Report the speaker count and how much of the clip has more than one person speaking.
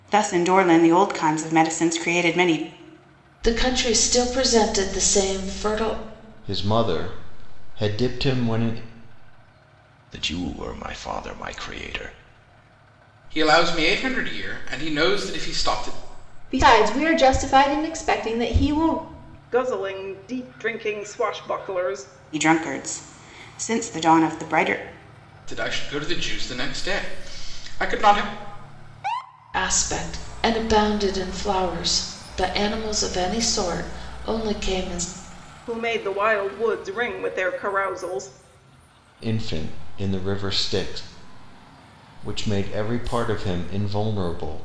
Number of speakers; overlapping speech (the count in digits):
7, no overlap